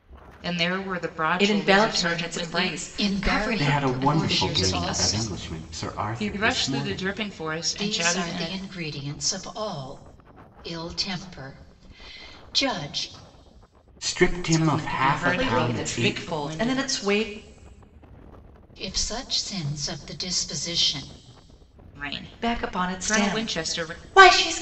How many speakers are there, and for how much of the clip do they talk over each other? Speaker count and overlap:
four, about 43%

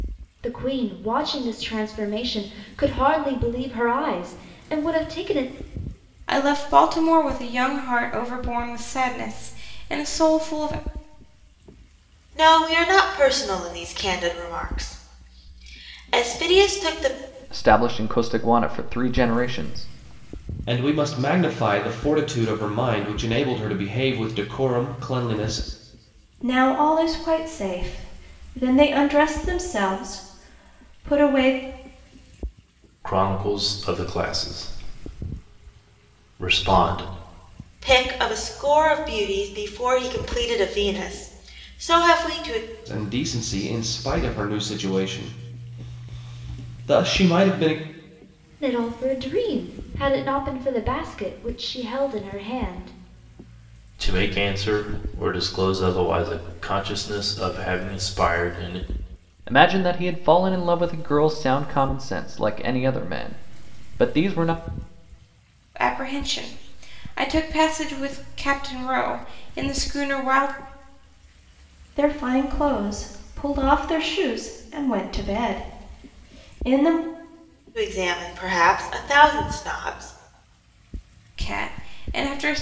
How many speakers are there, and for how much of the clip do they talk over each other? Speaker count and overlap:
seven, no overlap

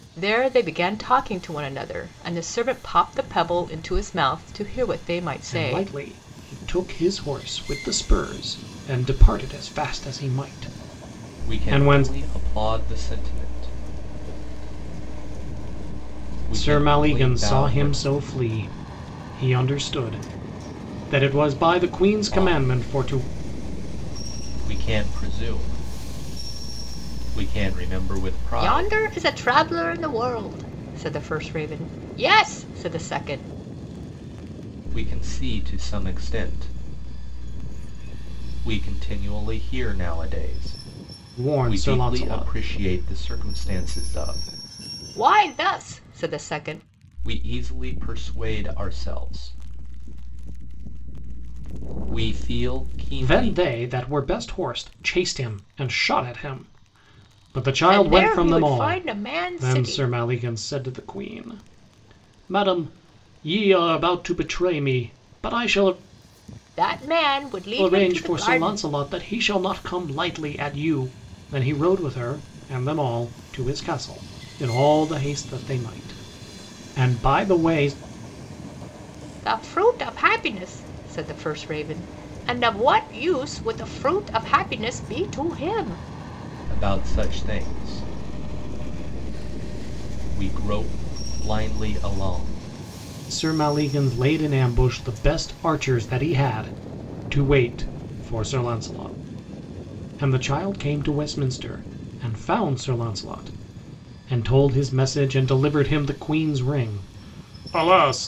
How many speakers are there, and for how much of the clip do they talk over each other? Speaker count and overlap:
three, about 7%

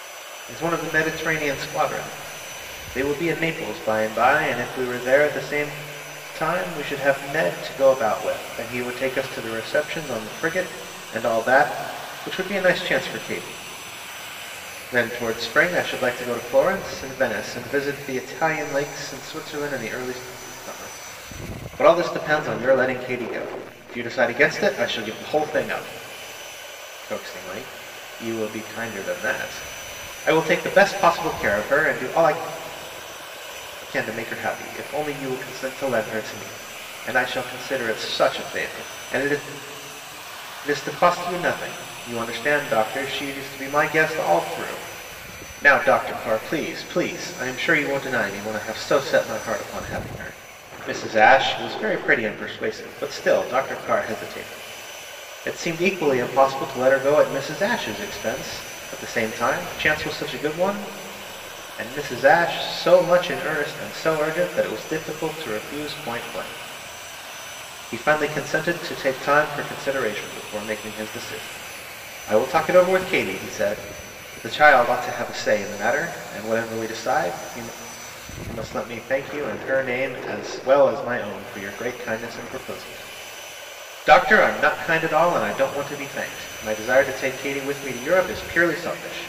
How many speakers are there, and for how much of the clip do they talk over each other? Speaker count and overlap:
one, no overlap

